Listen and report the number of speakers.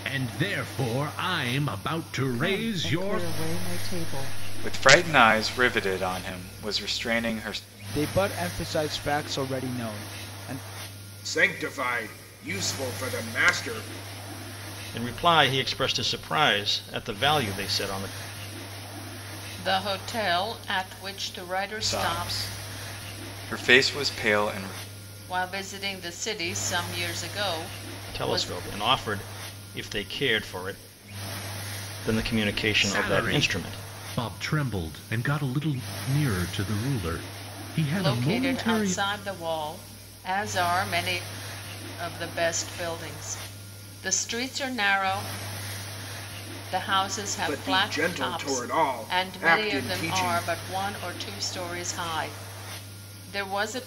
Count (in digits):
7